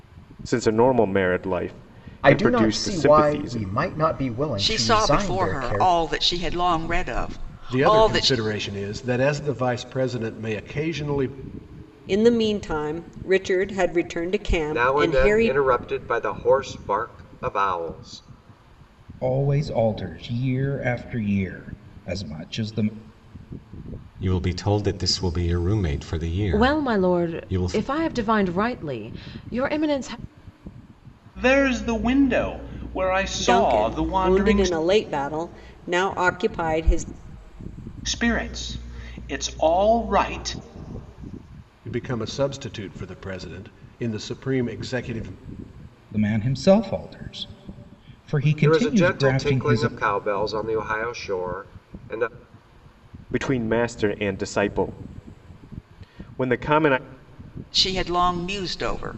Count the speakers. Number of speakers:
10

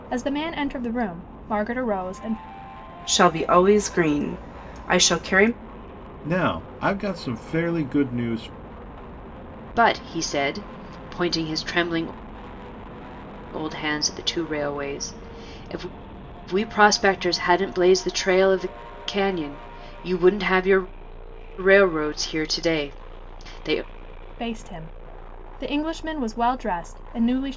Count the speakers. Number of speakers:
4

